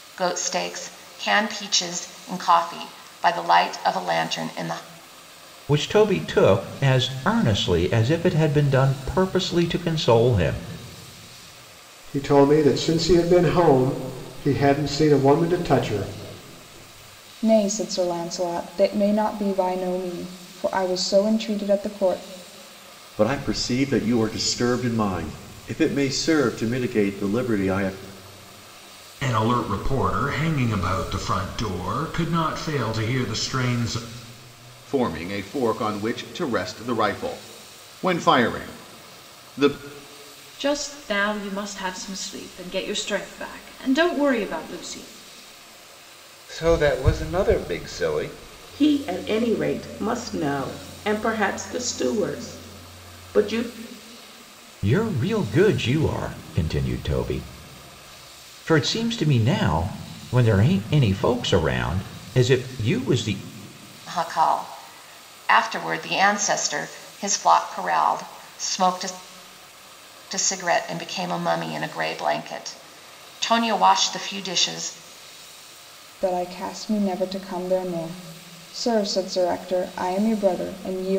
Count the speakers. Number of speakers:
10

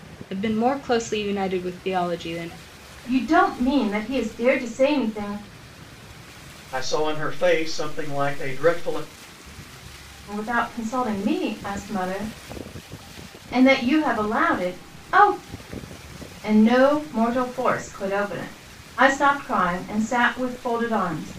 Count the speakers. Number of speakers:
3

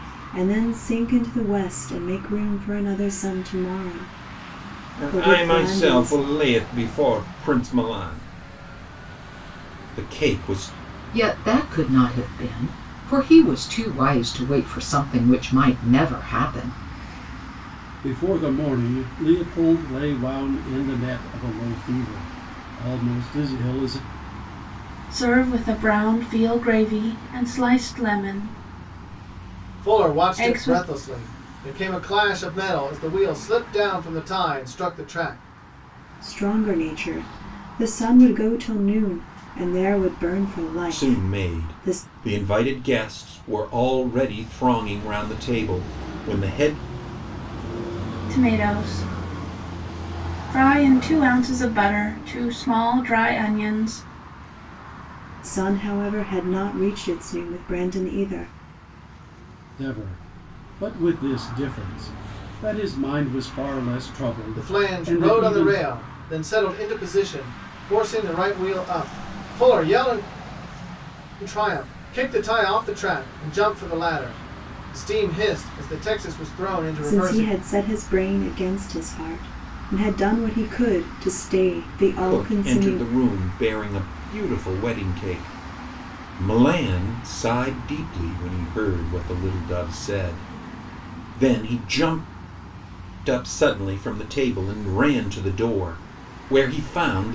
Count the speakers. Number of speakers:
6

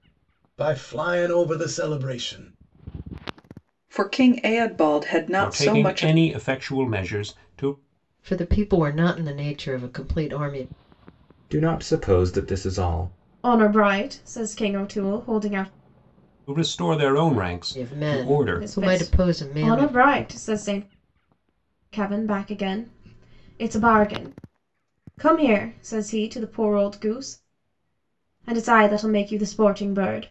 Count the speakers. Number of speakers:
6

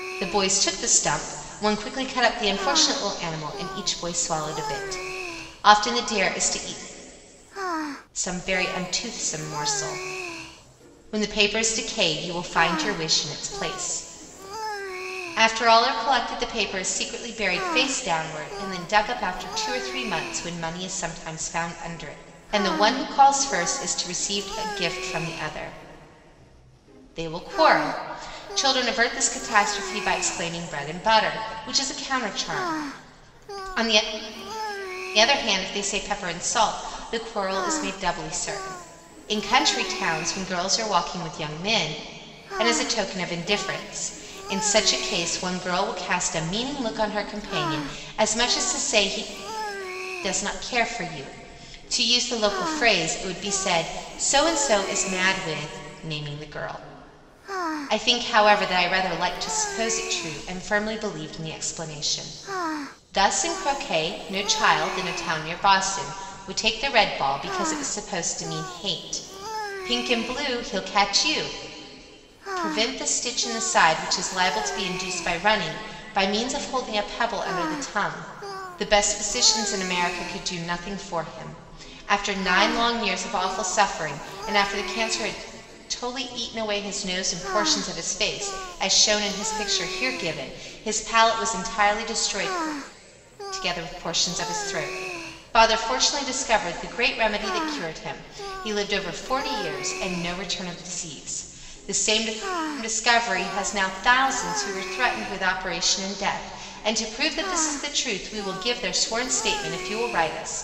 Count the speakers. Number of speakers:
1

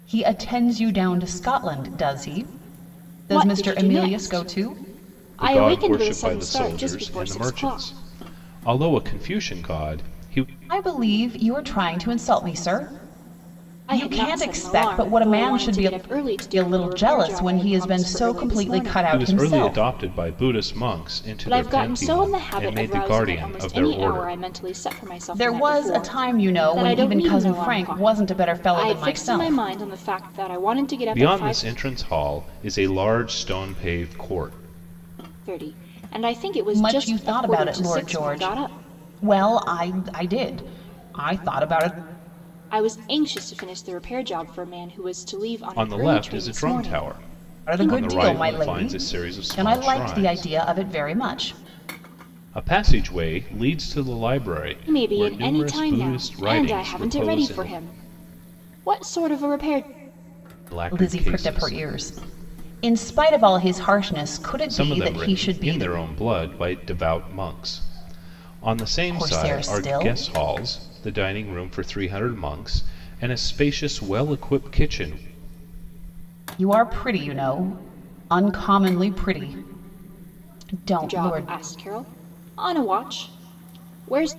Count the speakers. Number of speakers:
3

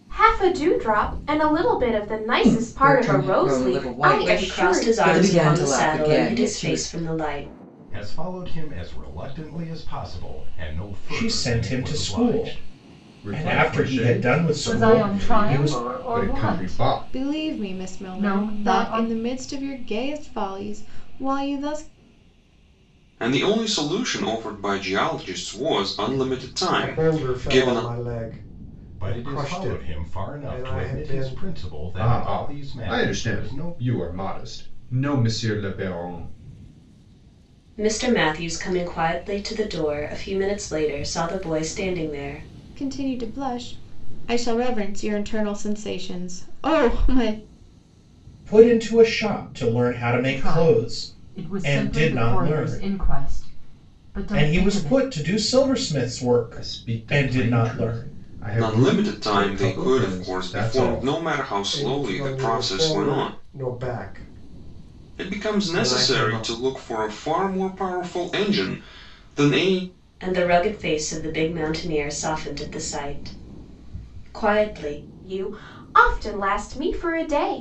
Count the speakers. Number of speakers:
10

